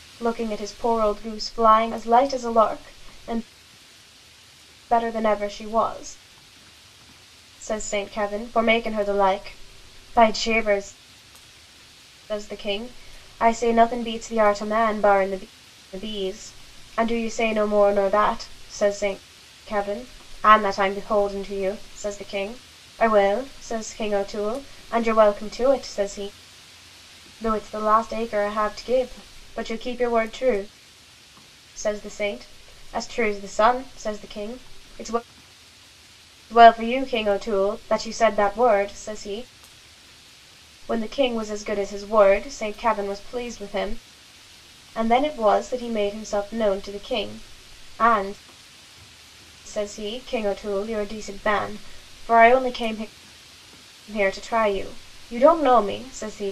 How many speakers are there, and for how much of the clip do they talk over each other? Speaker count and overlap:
1, no overlap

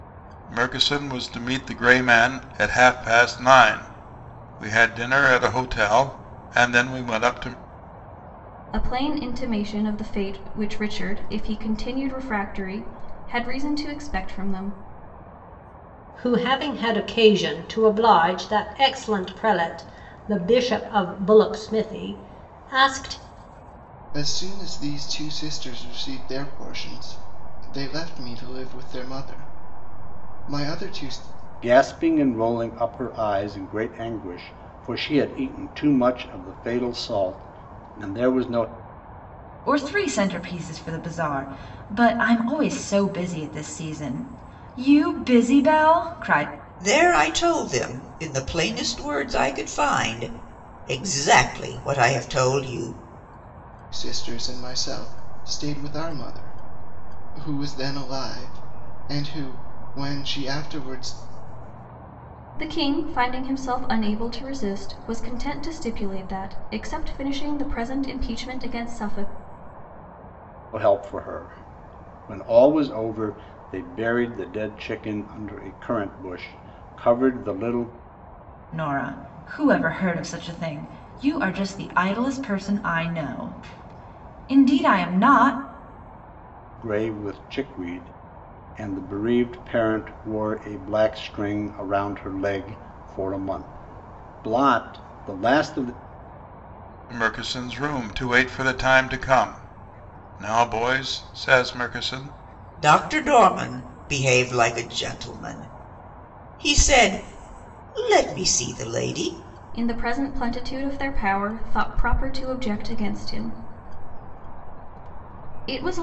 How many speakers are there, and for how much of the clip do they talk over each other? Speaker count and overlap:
7, no overlap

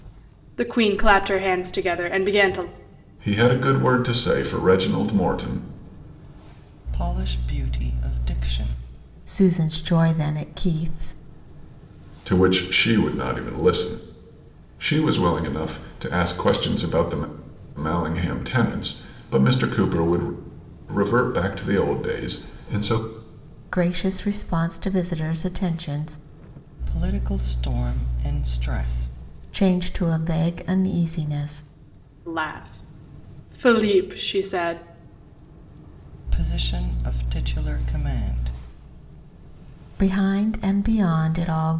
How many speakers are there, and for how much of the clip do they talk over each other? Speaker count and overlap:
4, no overlap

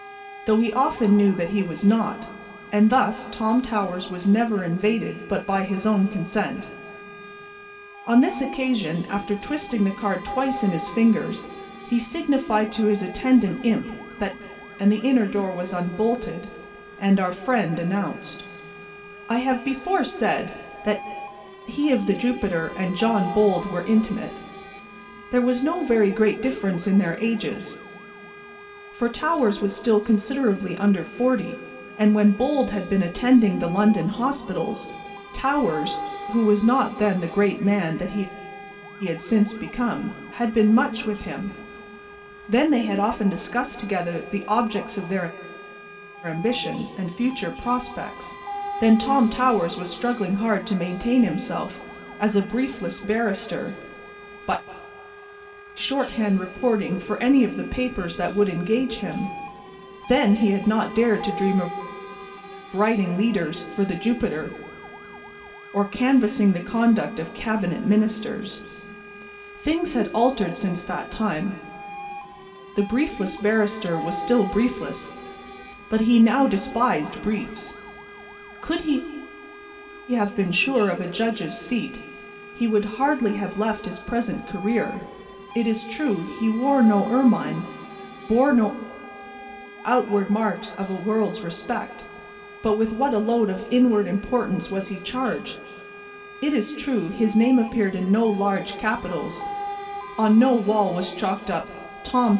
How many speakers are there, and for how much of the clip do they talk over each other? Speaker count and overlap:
1, no overlap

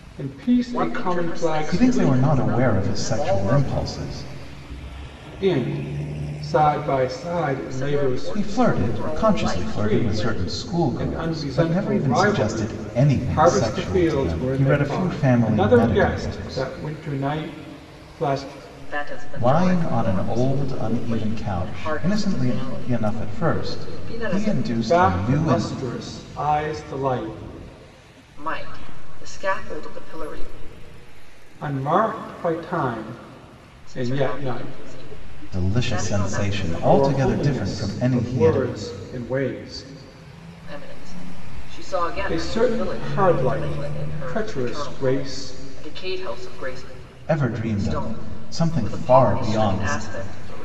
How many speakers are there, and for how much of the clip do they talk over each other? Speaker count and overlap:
3, about 53%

